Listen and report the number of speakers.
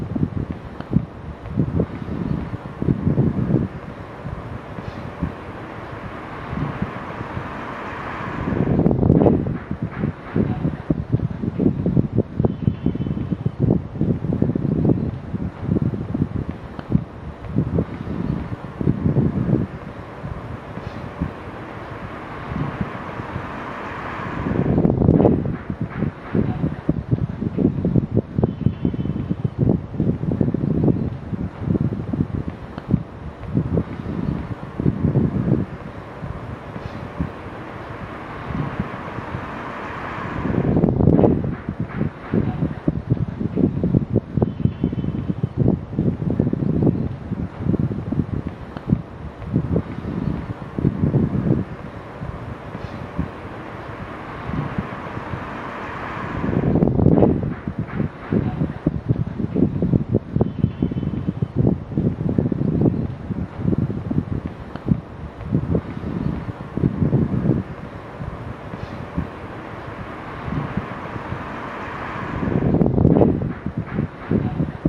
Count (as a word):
zero